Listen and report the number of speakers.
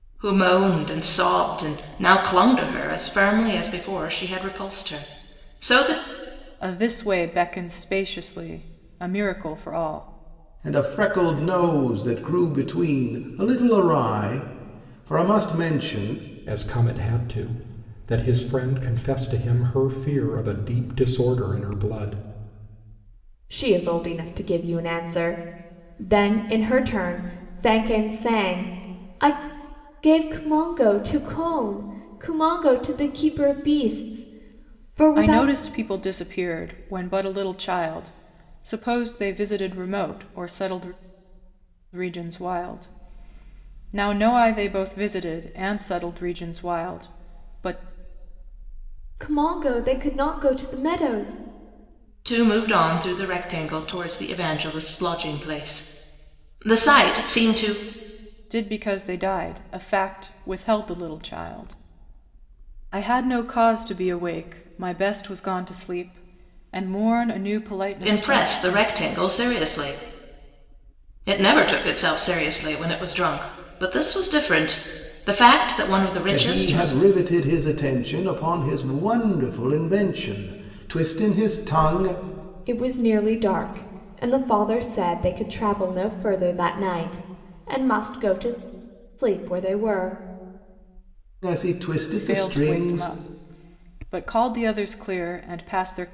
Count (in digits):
5